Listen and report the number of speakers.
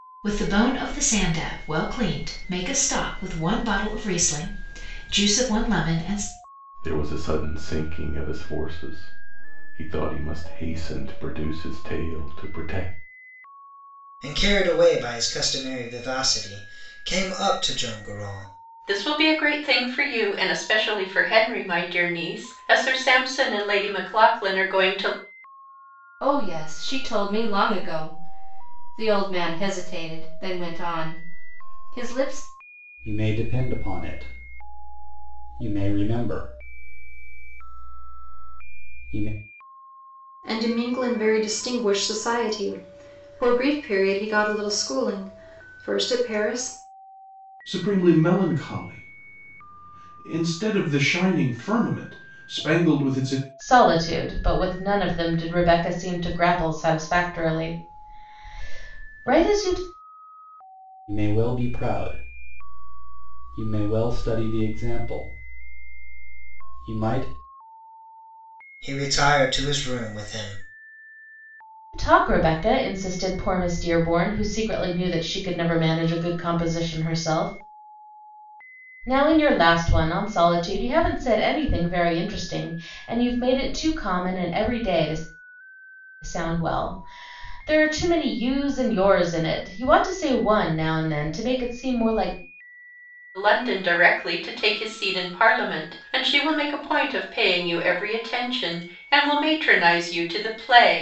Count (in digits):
9